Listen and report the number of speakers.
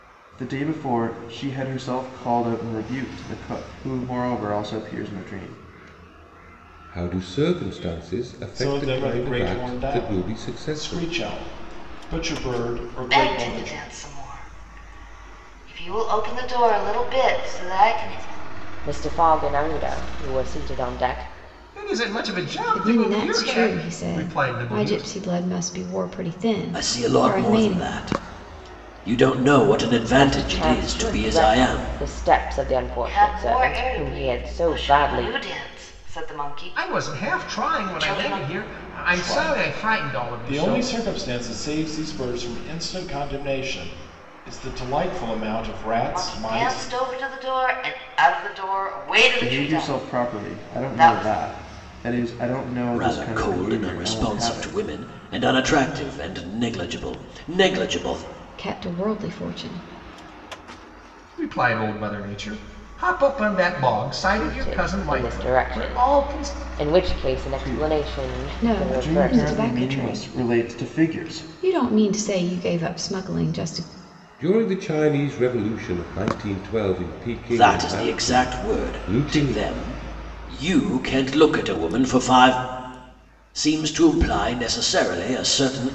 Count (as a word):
nine